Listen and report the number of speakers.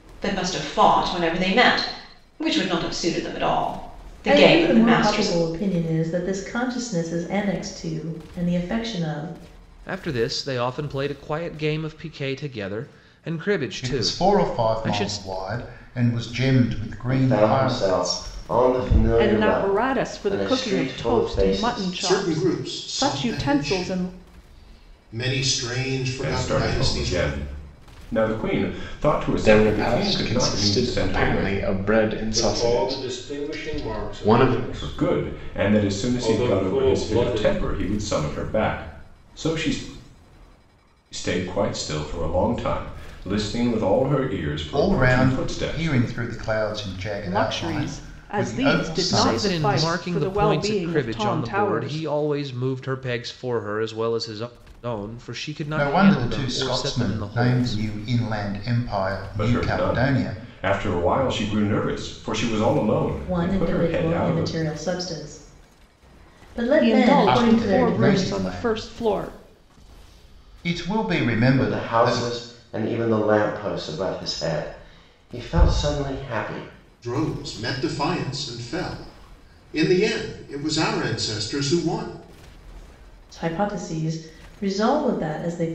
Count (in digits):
10